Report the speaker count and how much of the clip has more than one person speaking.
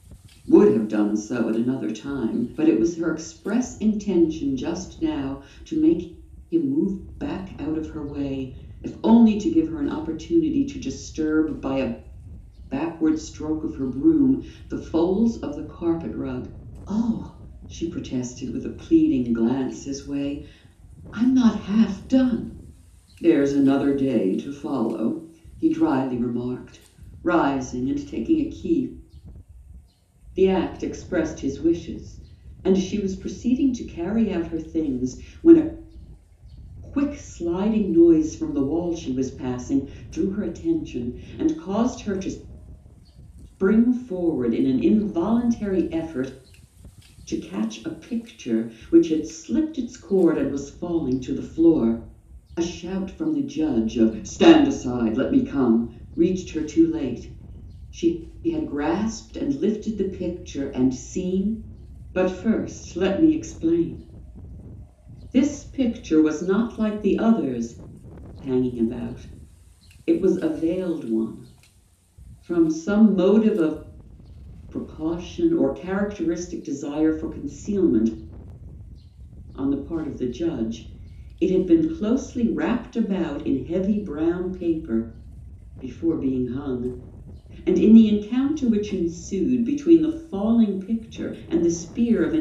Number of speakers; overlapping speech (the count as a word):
one, no overlap